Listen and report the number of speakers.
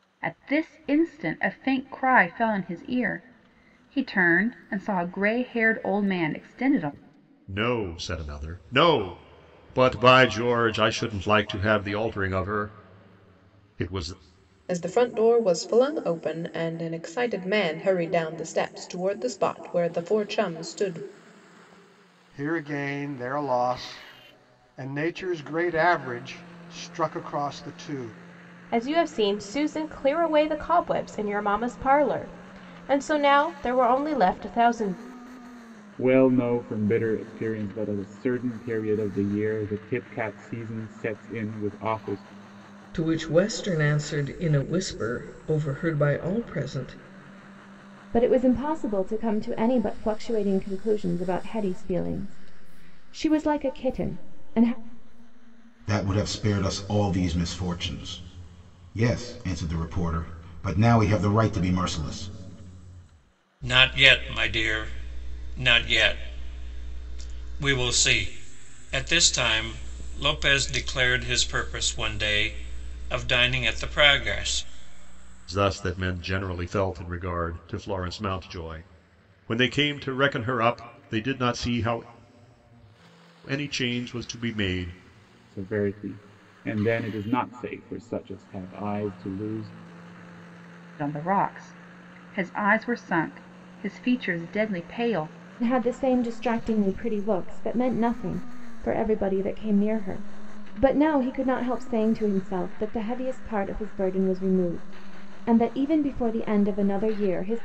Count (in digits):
10